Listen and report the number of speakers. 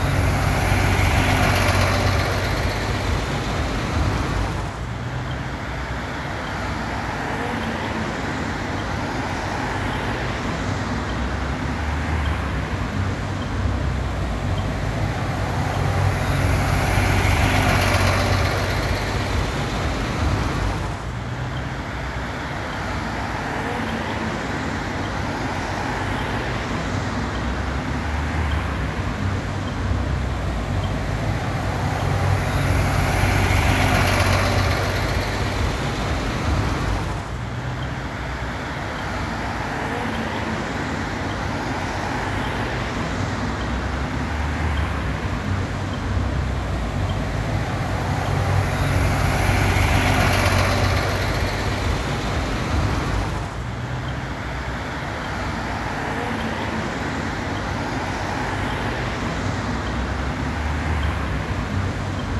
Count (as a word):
zero